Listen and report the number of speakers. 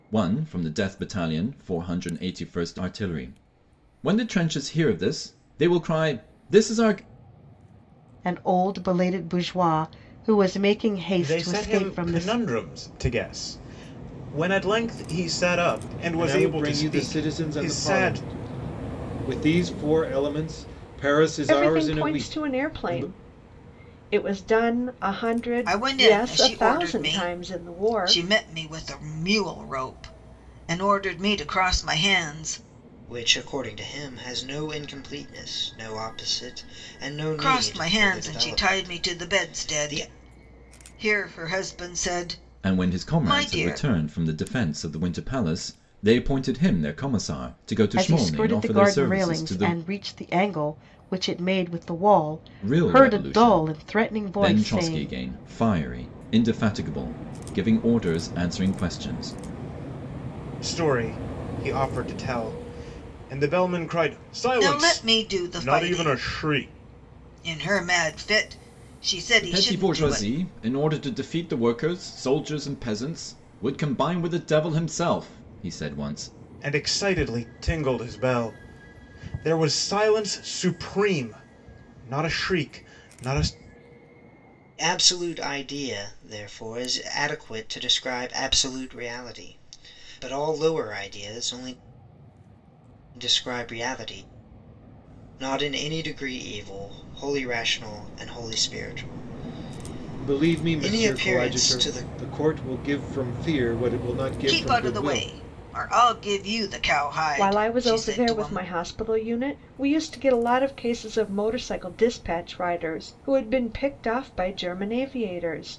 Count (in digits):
7